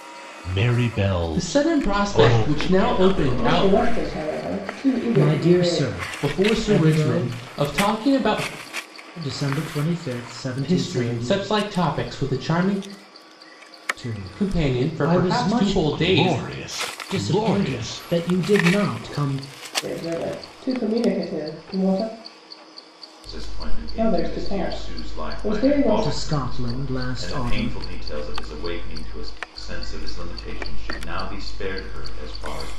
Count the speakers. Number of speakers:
five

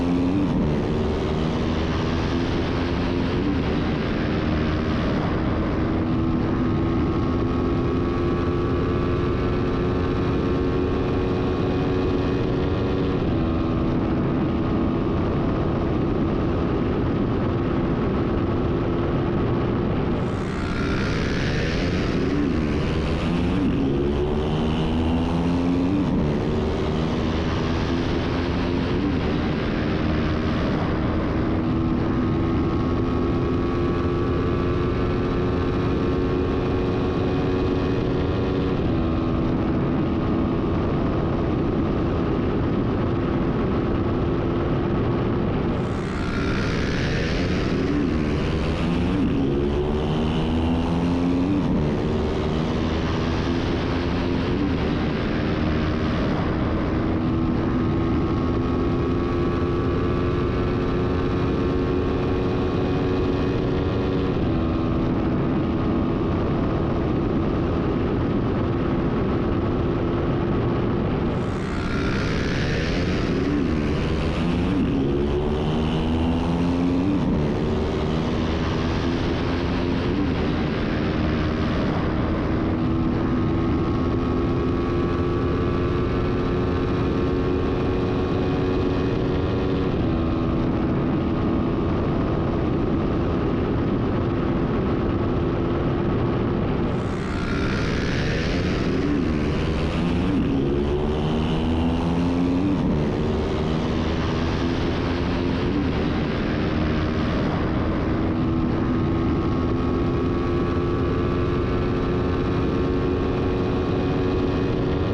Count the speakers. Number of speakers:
zero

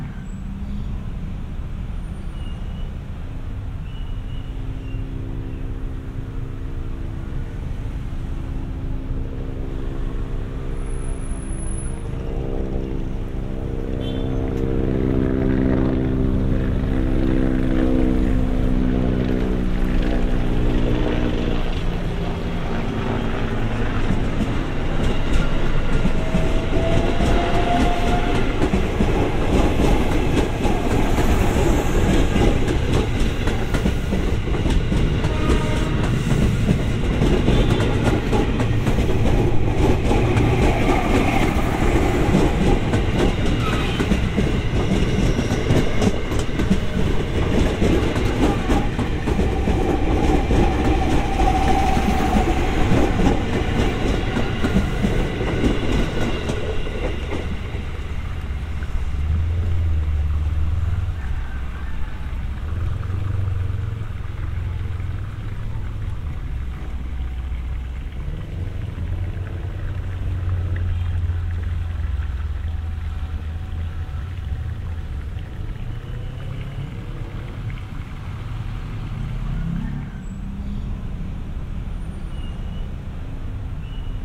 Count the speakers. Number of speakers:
zero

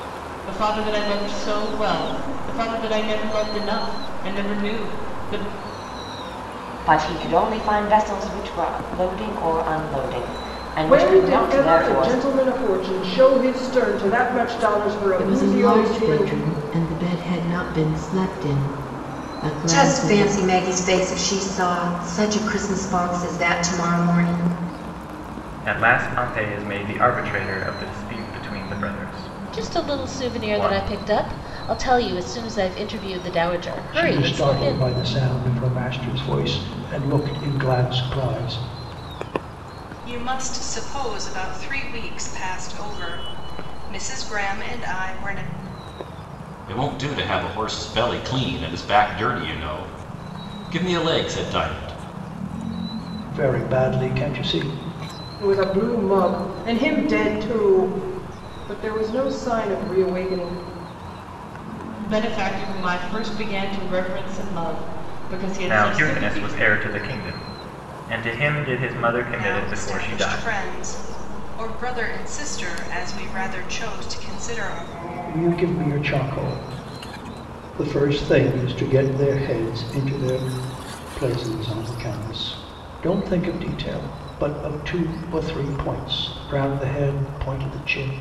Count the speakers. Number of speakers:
ten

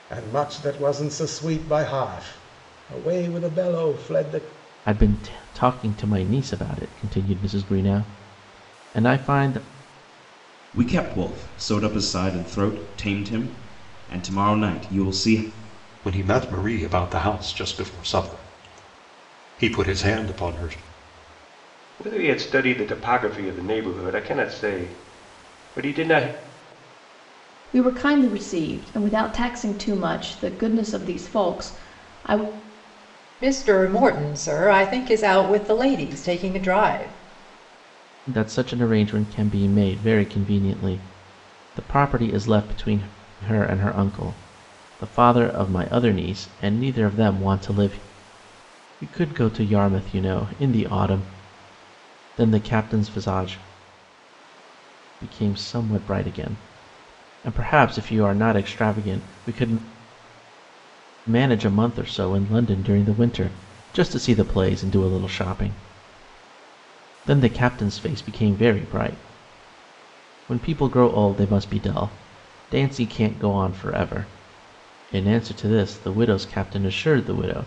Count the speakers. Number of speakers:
seven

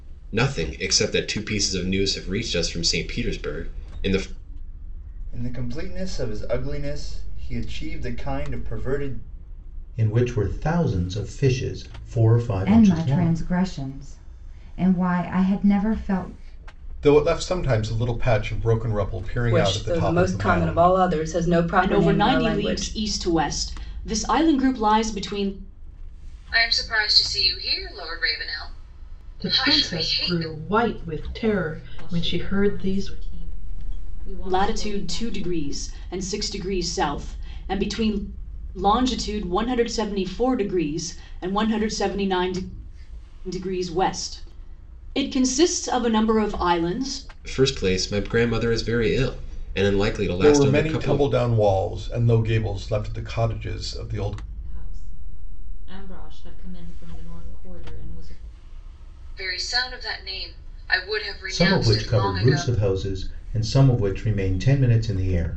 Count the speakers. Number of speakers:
ten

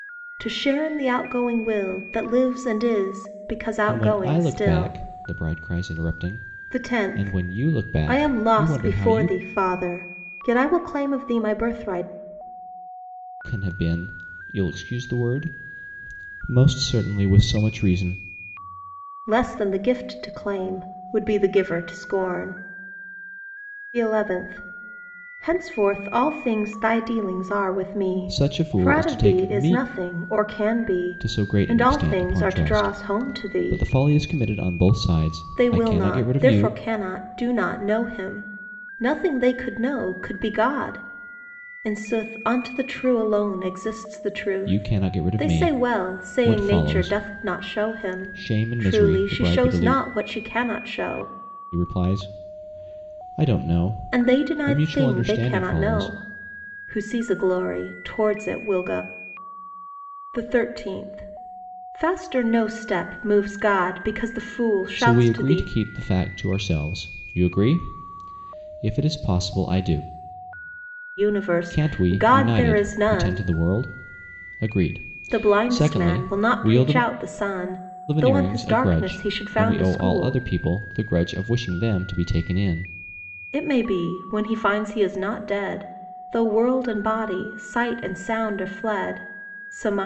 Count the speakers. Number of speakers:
two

